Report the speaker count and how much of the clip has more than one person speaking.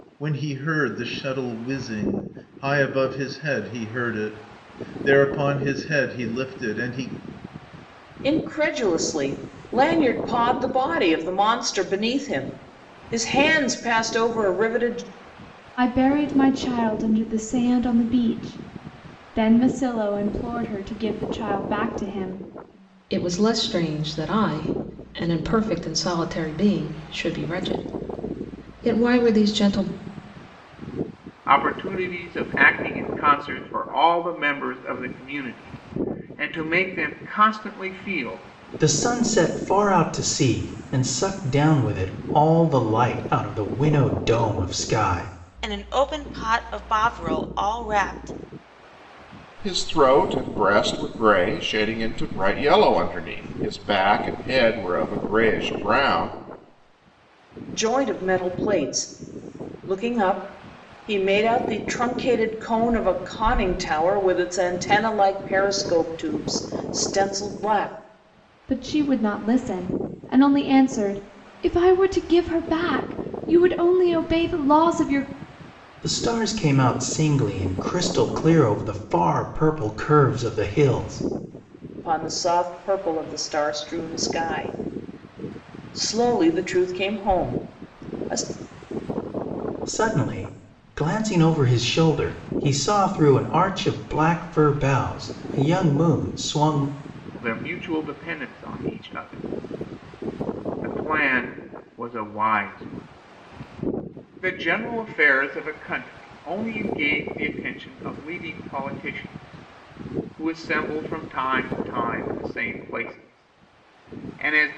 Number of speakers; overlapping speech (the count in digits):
8, no overlap